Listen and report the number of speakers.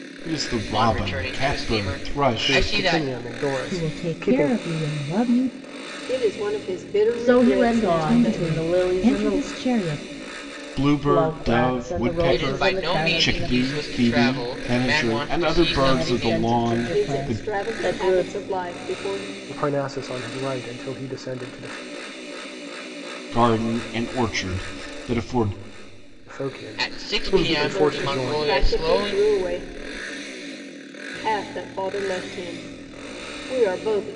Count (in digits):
6